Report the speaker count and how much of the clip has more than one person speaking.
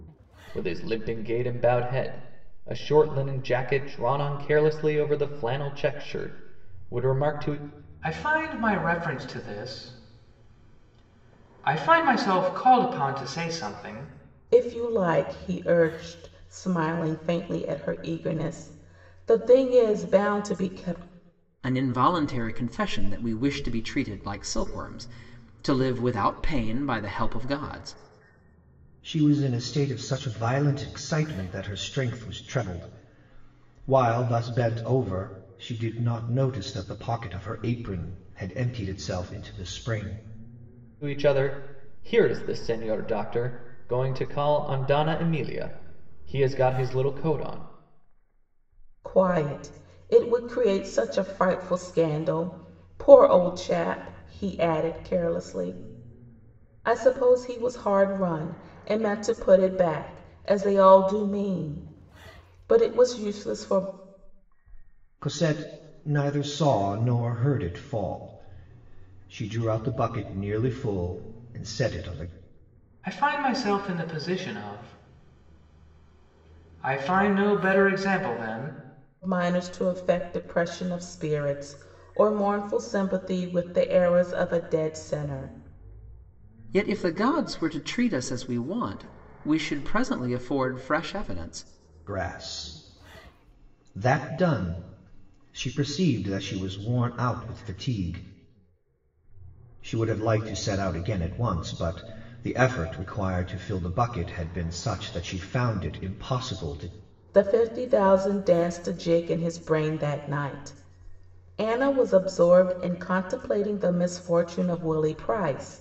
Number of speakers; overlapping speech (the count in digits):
5, no overlap